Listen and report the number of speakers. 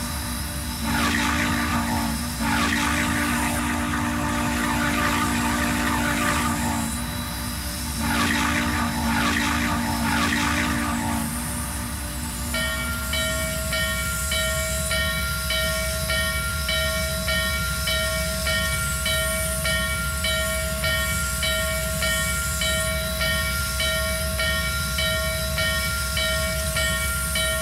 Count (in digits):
0